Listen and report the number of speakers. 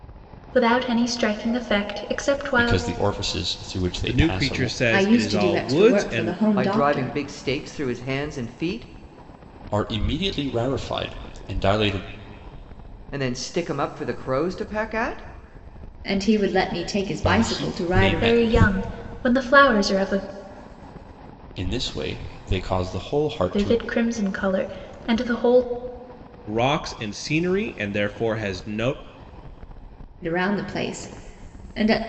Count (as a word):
five